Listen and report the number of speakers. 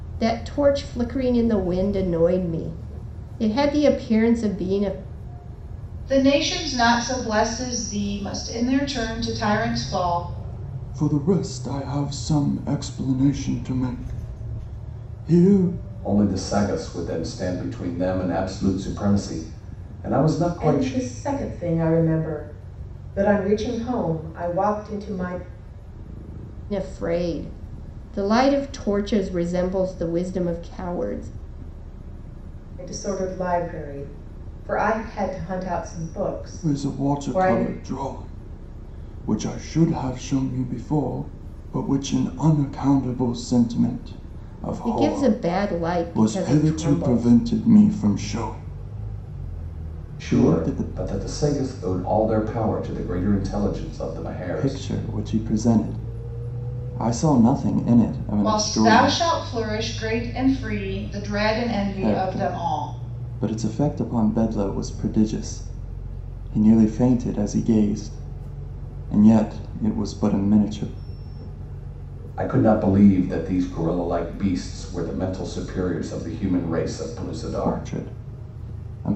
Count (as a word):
five